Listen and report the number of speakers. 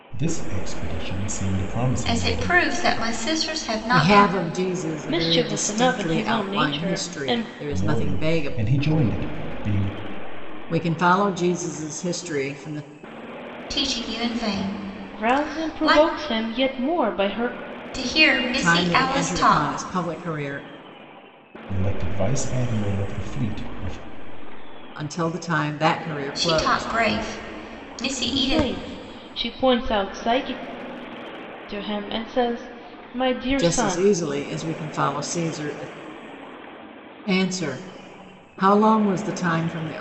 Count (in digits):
4